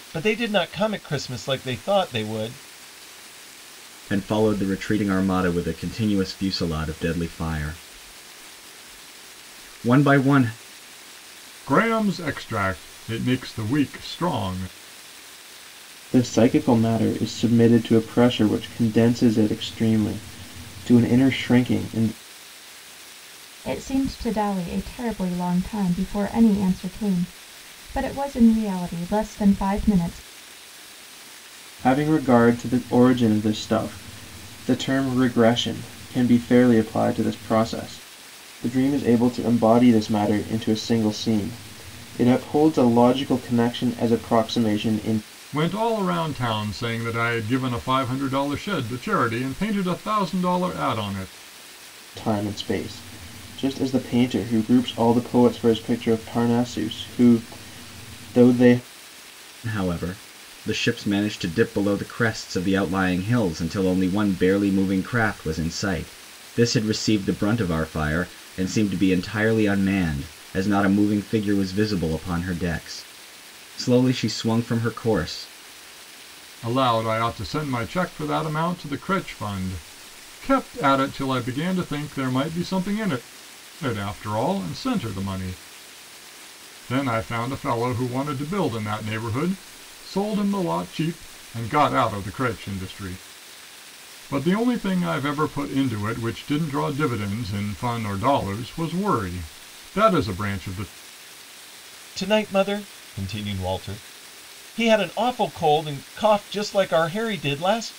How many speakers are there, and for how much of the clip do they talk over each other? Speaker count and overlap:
5, no overlap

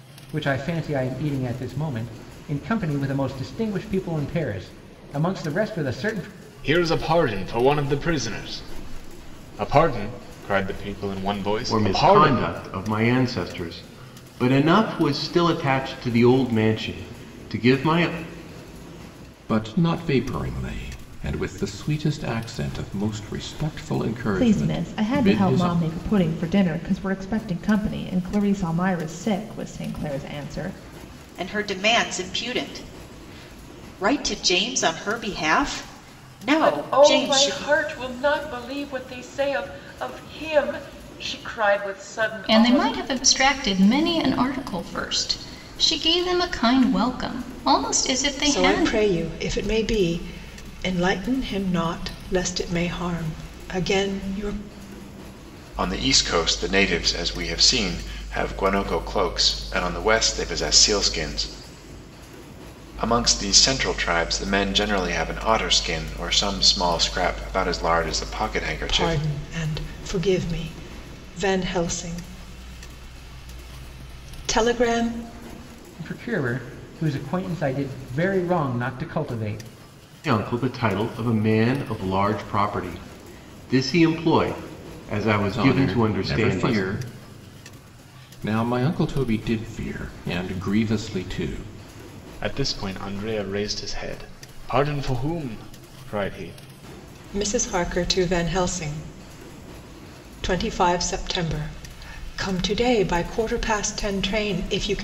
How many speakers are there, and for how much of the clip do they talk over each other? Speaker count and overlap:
10, about 6%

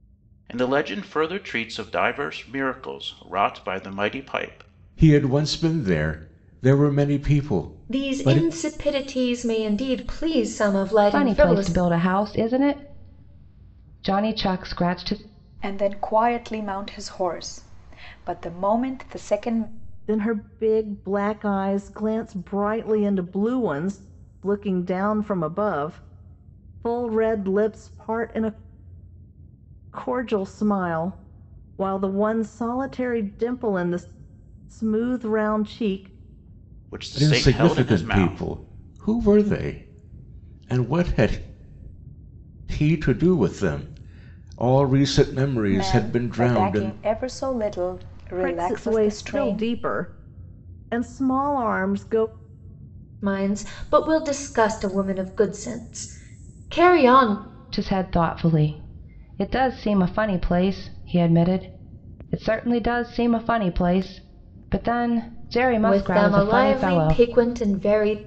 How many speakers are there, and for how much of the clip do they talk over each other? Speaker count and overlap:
6, about 10%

